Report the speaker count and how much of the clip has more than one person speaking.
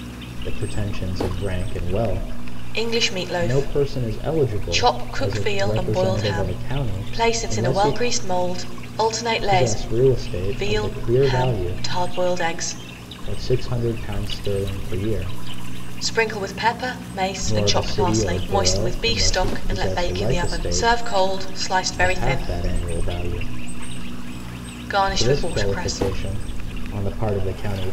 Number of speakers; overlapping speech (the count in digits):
2, about 41%